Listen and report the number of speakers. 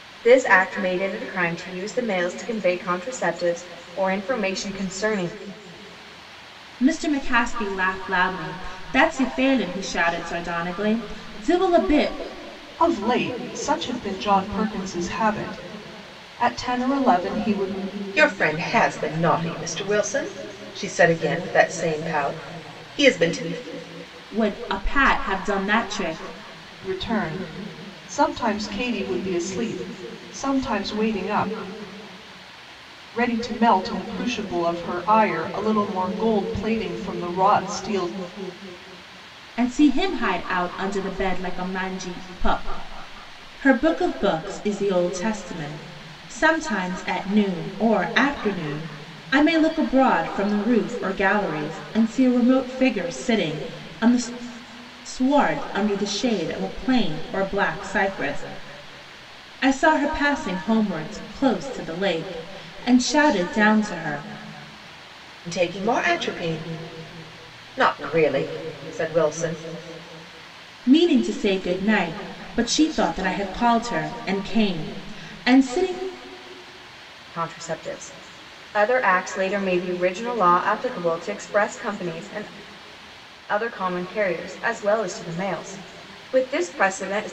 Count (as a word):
four